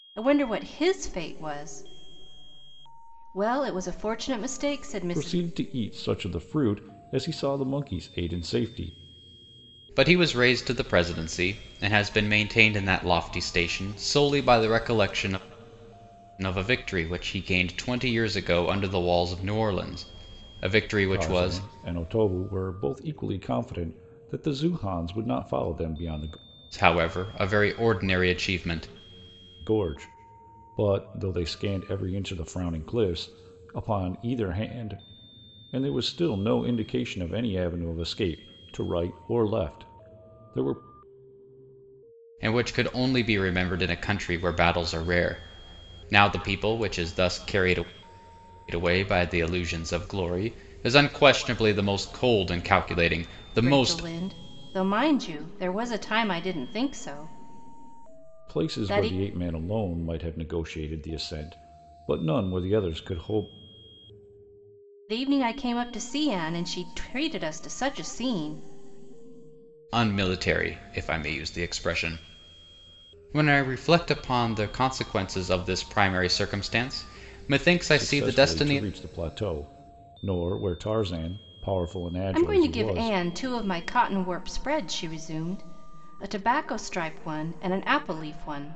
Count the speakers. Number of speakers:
three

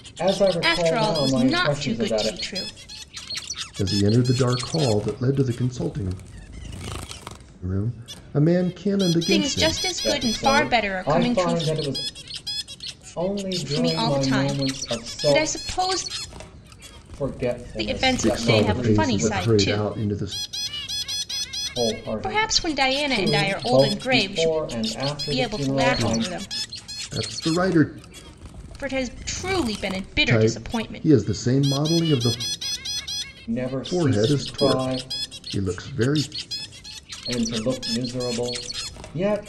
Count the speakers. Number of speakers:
three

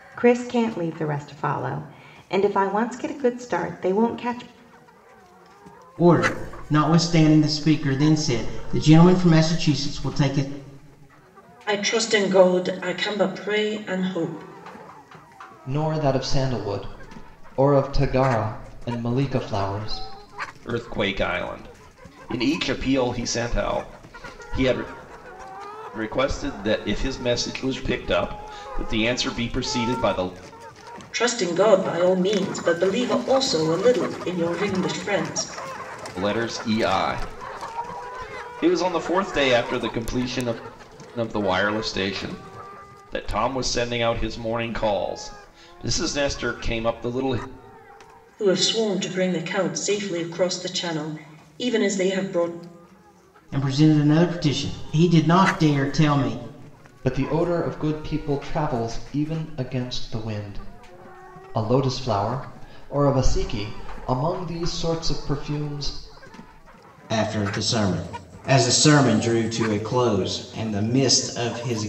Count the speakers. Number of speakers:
five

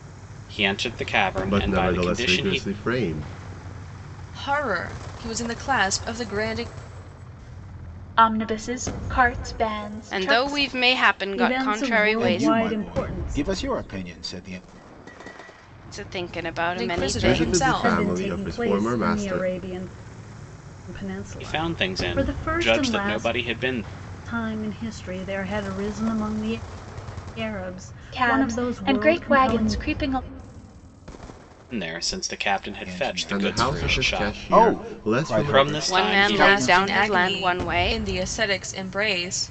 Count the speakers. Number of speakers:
seven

